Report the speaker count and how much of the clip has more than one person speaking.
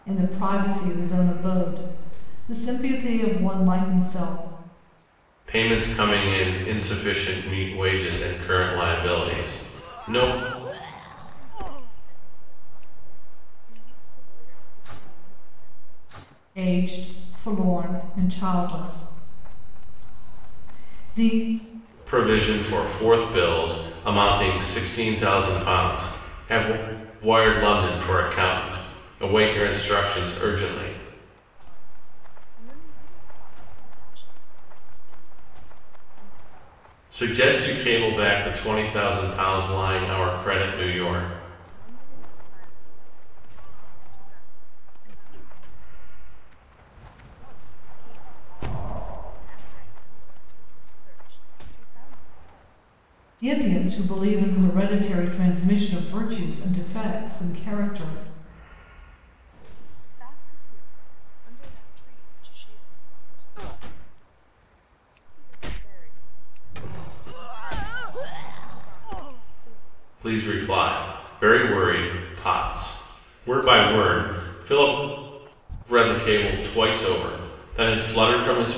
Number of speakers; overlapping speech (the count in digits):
3, no overlap